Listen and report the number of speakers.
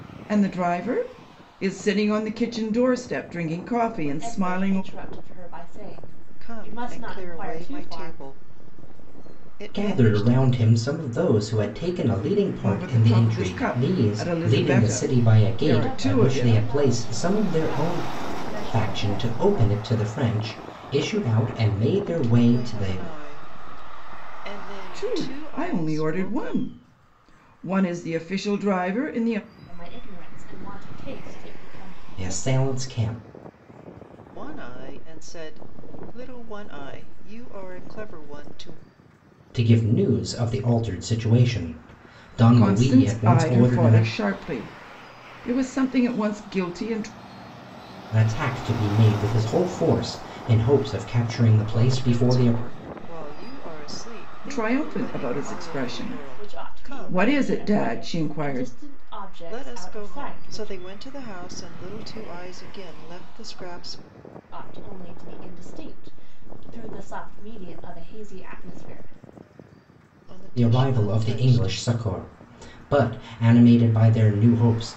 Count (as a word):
four